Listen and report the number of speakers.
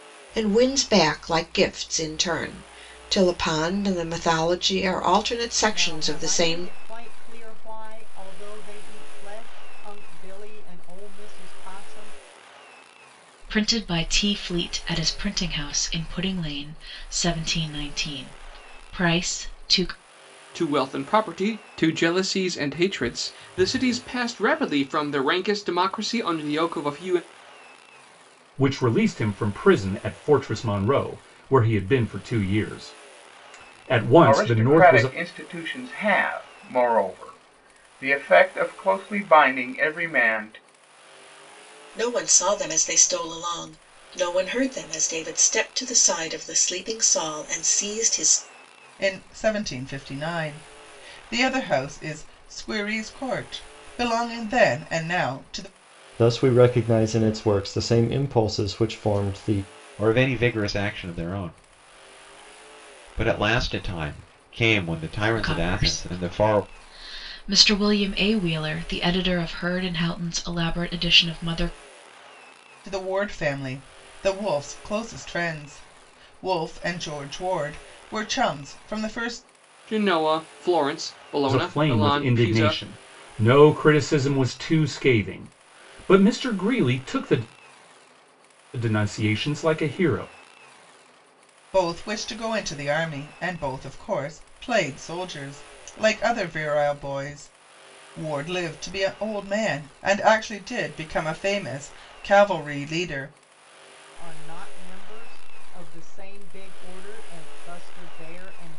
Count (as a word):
ten